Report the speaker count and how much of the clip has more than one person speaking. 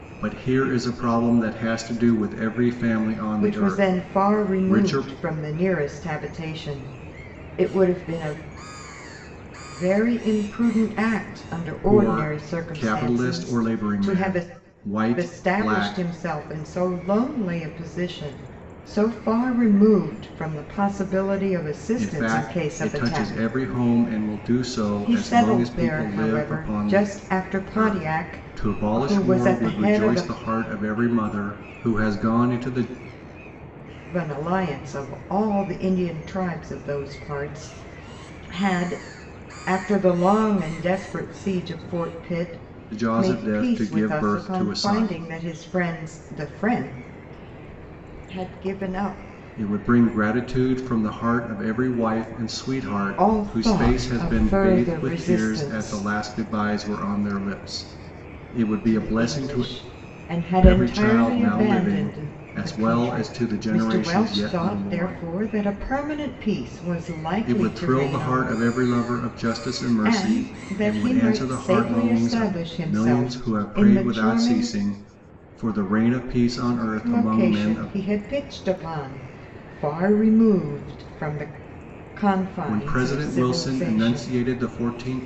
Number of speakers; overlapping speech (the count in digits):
2, about 35%